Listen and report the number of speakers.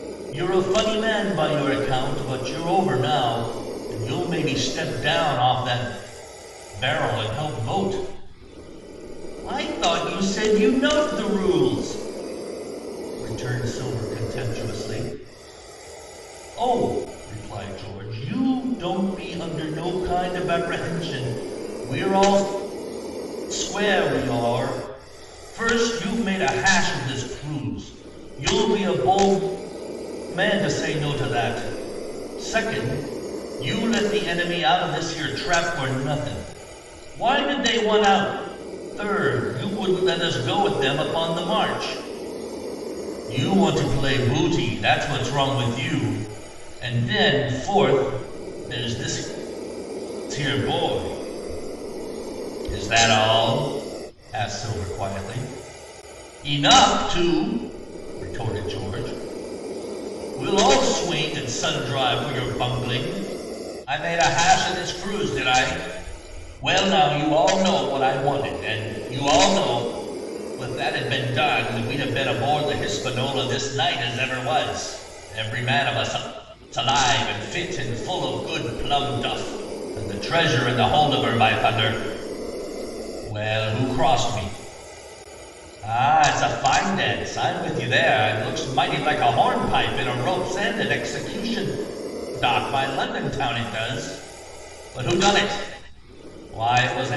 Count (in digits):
1